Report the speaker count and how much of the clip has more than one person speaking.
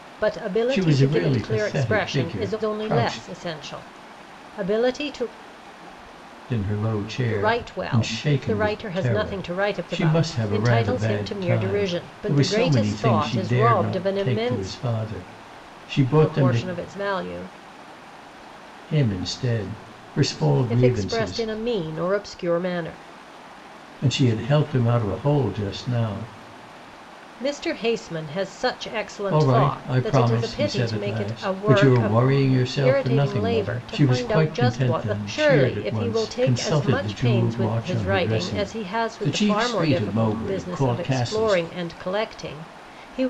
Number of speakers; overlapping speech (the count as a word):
two, about 53%